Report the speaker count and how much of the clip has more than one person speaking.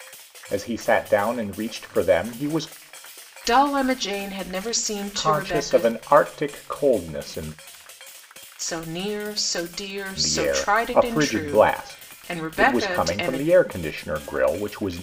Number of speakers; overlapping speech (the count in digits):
2, about 24%